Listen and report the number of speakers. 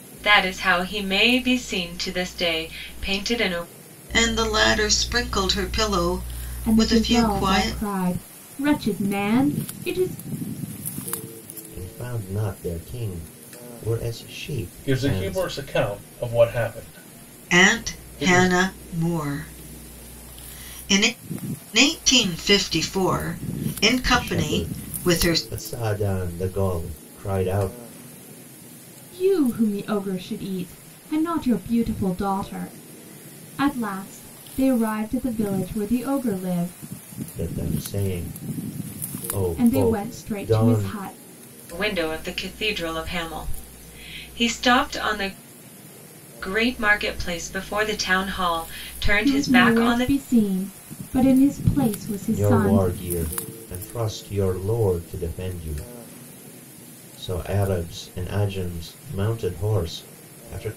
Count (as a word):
five